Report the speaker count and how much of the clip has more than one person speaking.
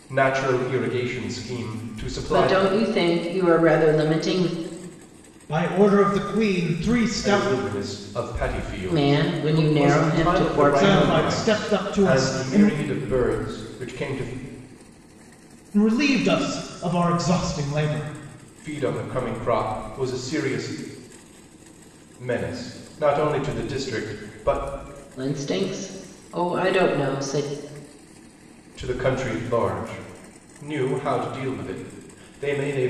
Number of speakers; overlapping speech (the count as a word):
three, about 12%